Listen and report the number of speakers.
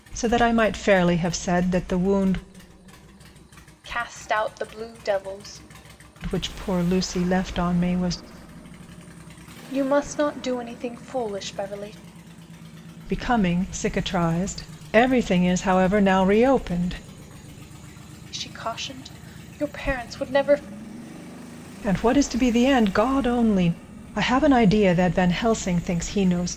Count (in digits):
2